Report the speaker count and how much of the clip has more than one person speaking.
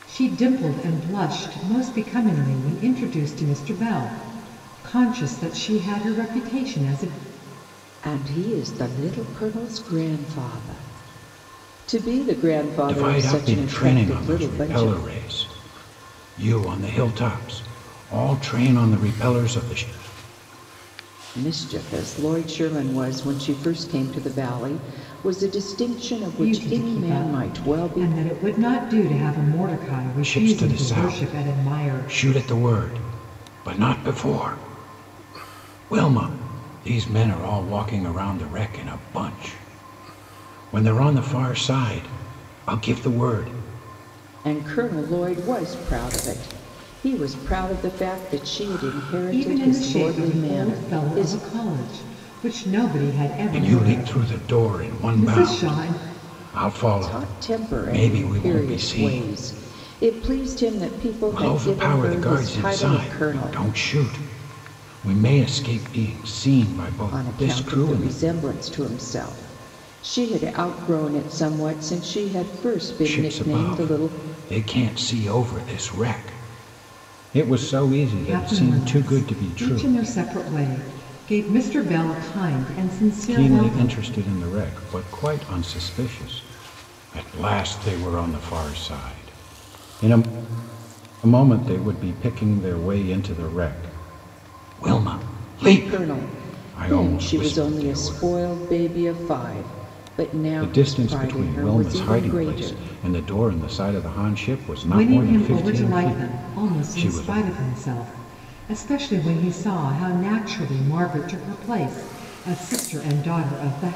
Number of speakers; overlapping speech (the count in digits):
3, about 24%